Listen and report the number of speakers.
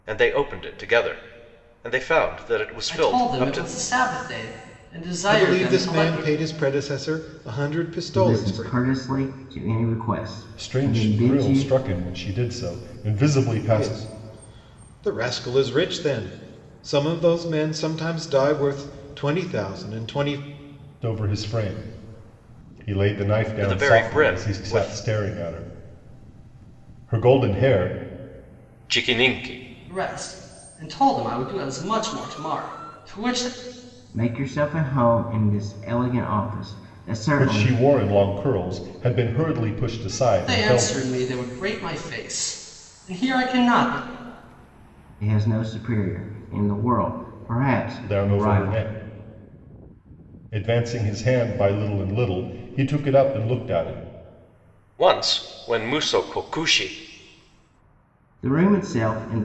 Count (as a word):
five